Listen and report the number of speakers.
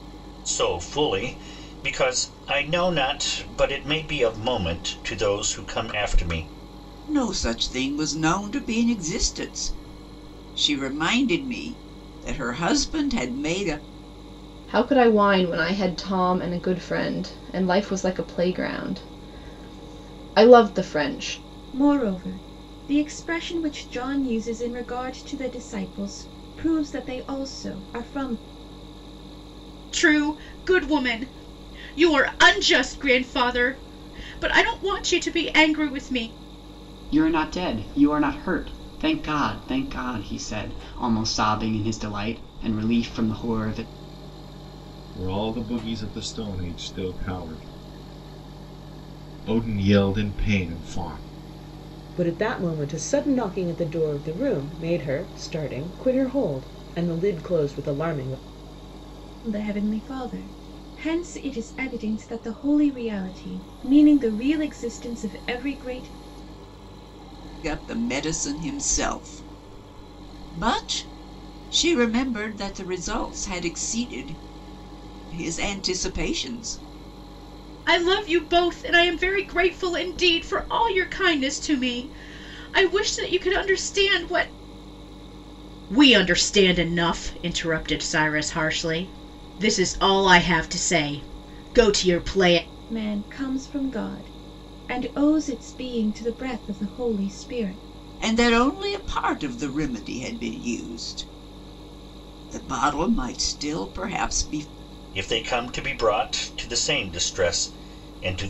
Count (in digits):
8